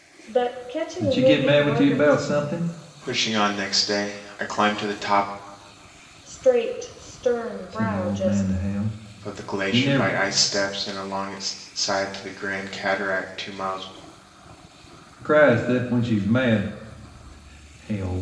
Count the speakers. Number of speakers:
three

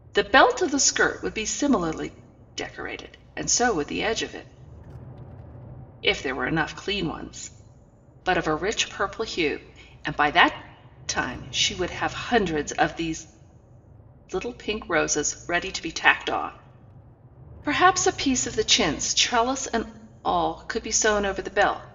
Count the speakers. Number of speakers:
one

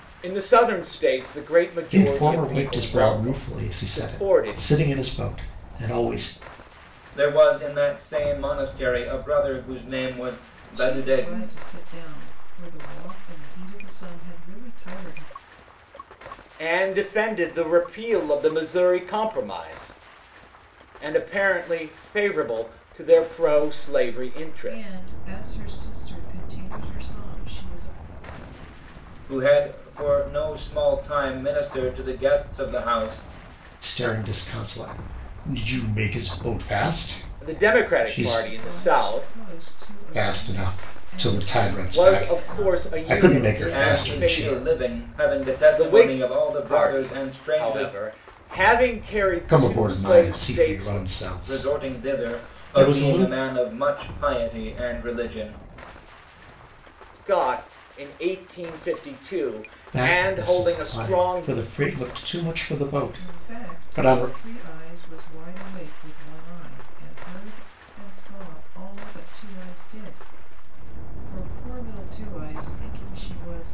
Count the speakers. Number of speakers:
four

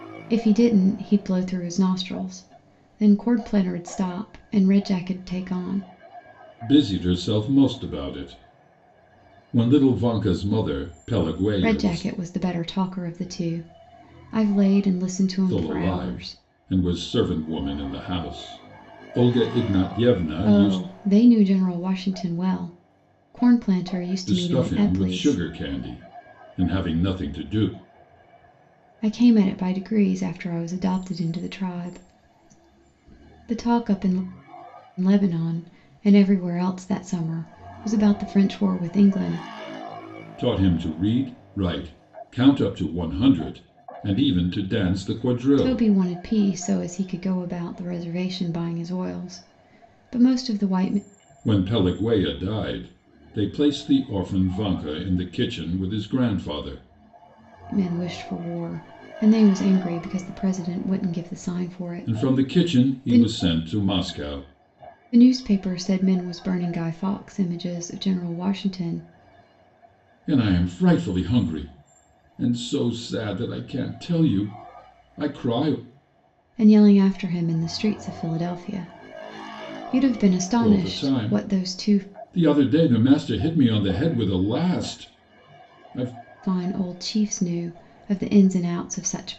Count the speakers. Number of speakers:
two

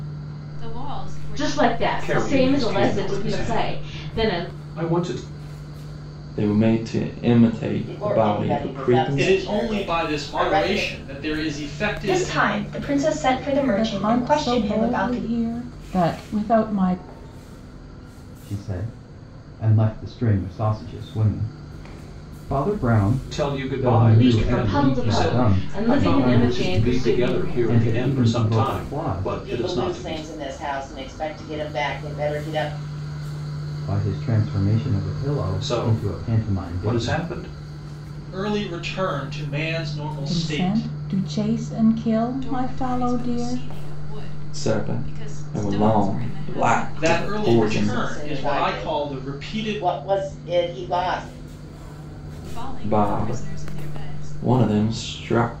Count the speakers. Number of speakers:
nine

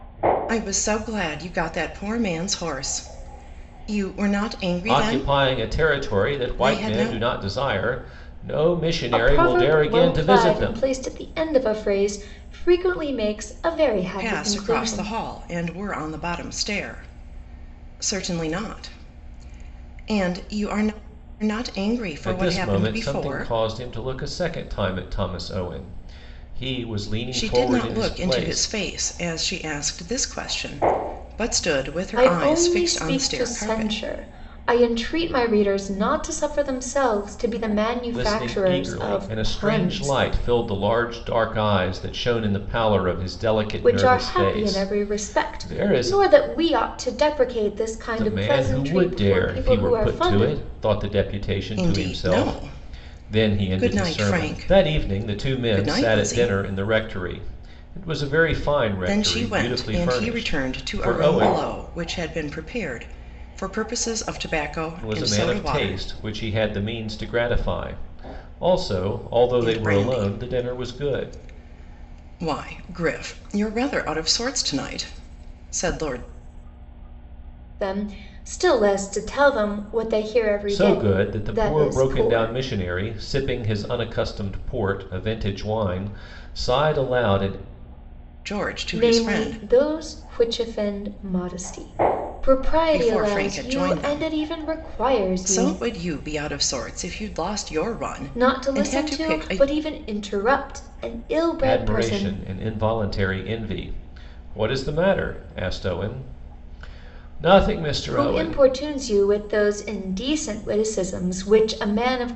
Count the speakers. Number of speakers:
three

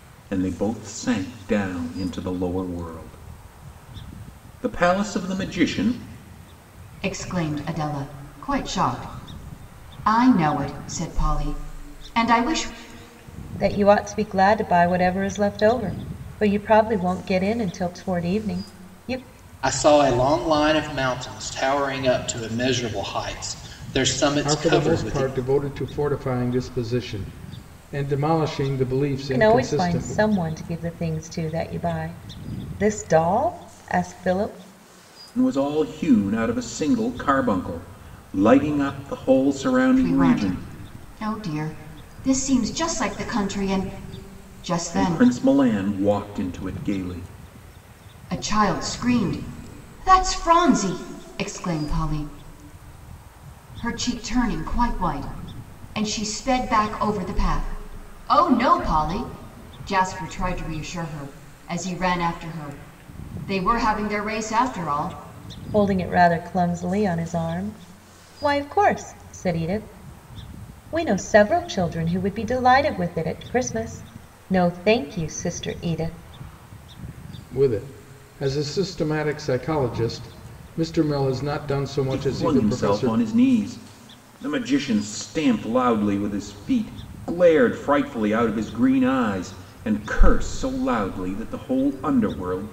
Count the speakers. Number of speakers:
five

